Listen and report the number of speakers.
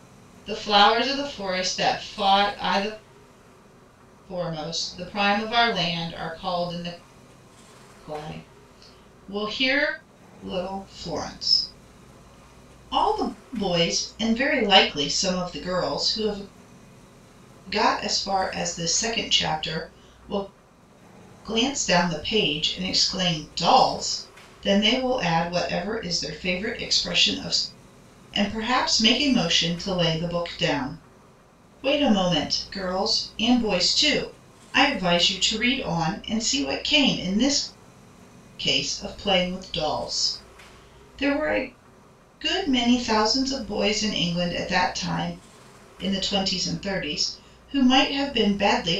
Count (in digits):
1